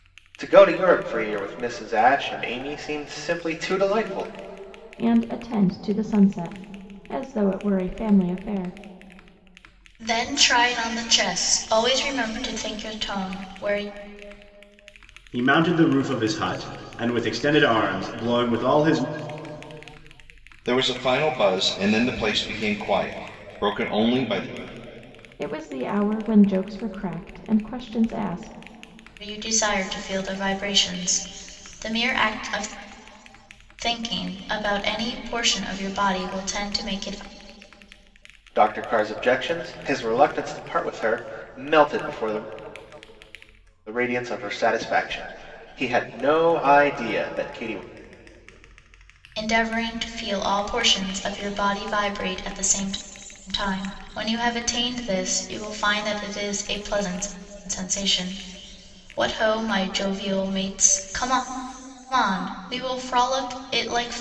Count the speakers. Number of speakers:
five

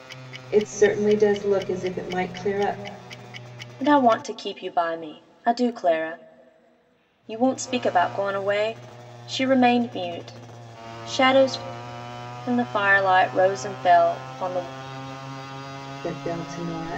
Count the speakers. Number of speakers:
two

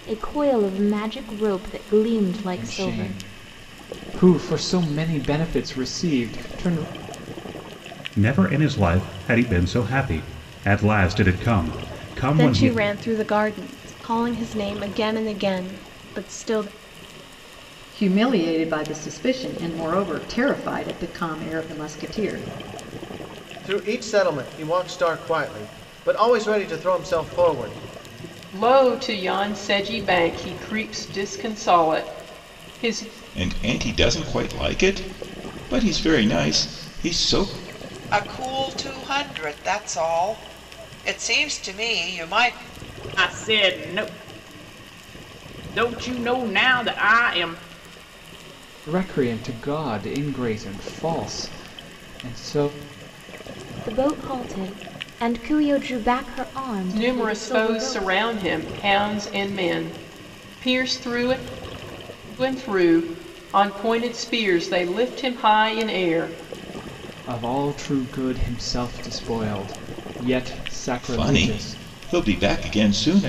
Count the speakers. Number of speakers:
ten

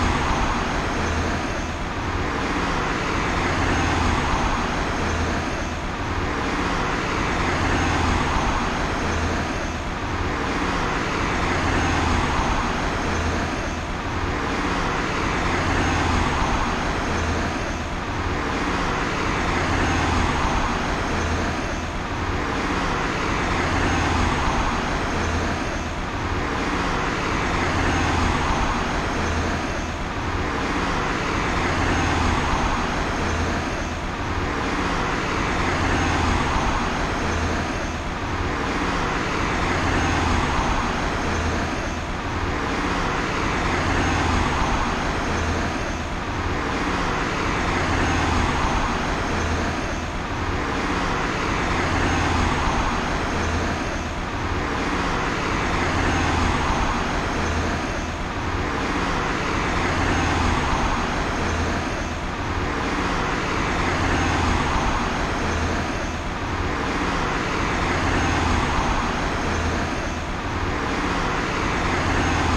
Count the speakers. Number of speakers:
zero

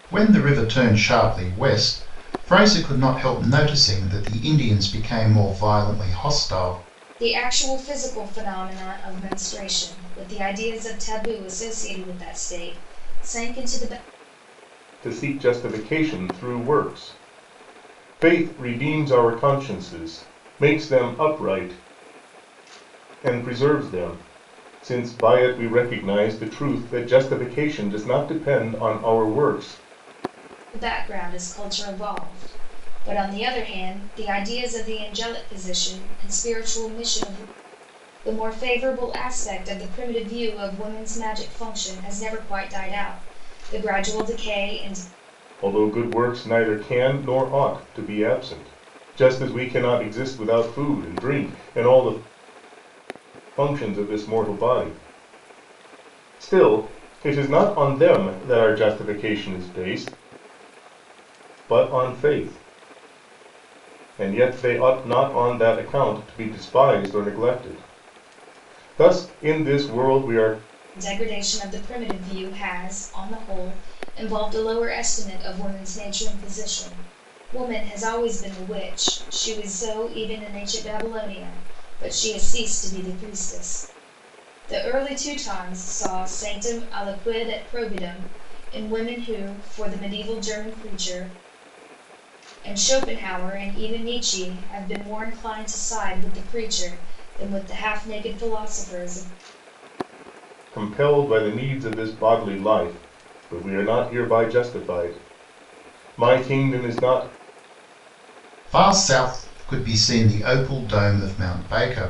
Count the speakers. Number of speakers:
three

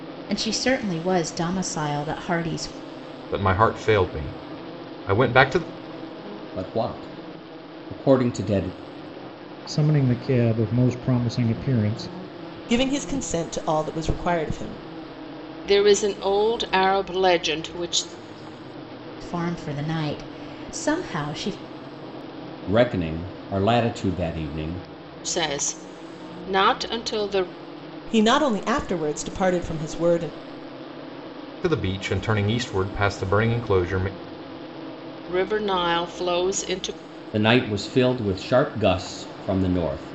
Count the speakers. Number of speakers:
six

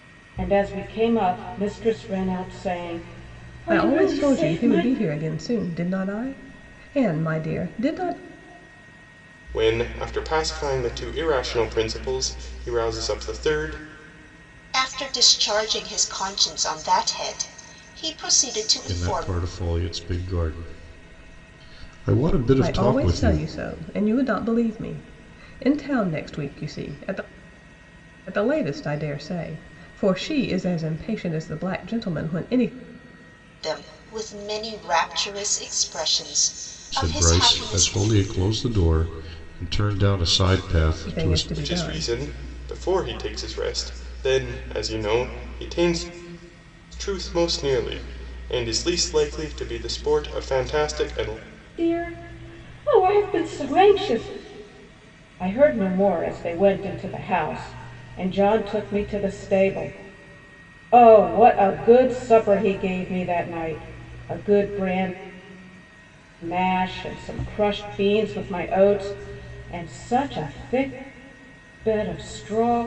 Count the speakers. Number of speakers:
five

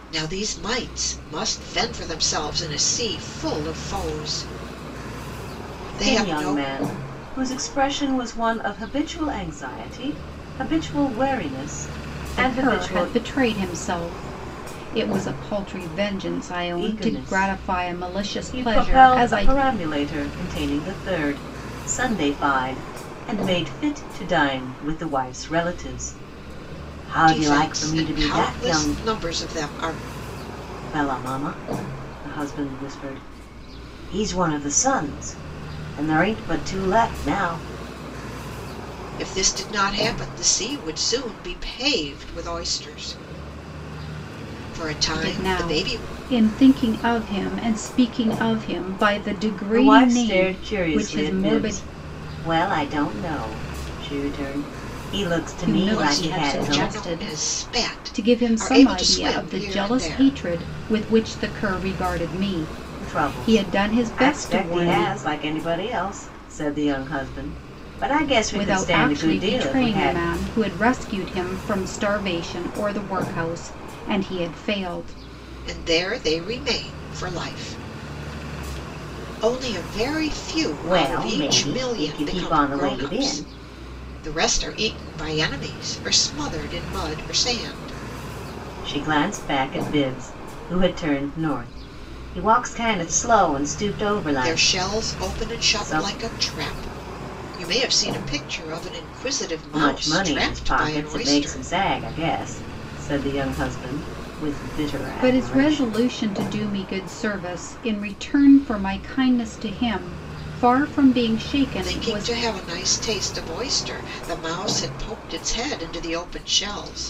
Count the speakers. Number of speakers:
three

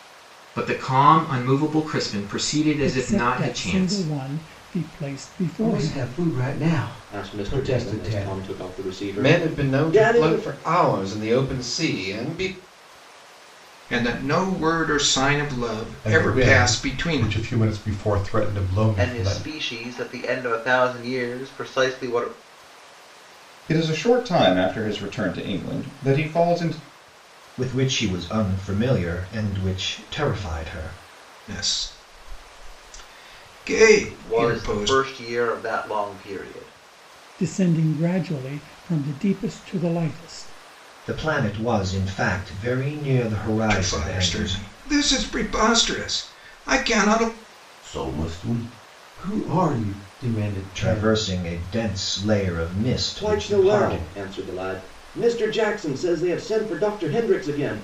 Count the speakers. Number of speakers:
ten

